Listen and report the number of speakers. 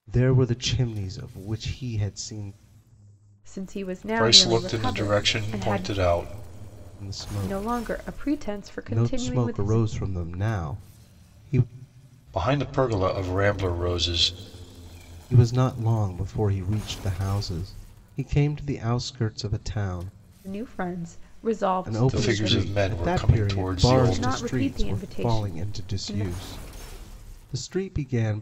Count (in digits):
3